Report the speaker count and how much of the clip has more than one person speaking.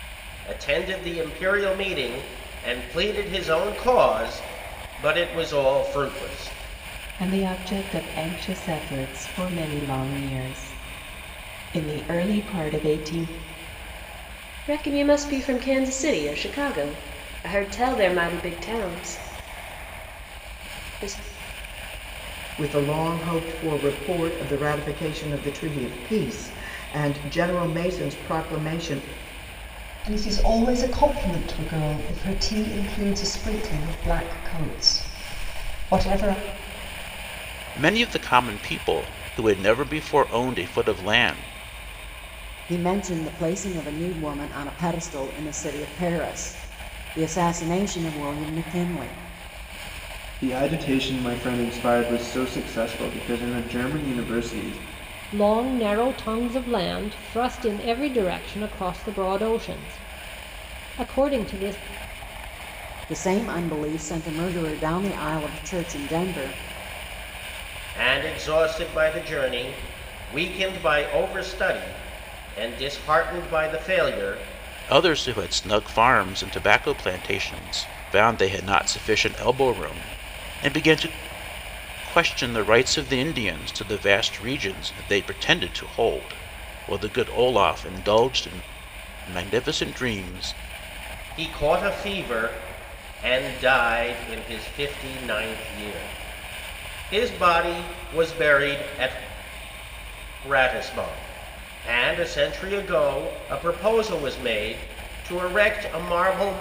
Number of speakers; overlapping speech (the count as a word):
nine, no overlap